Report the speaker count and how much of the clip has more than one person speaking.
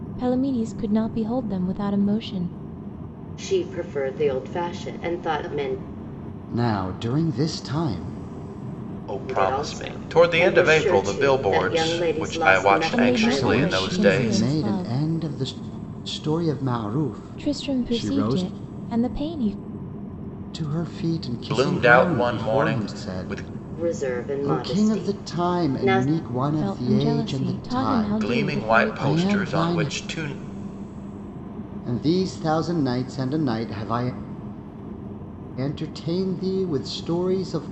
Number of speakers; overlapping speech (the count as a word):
four, about 39%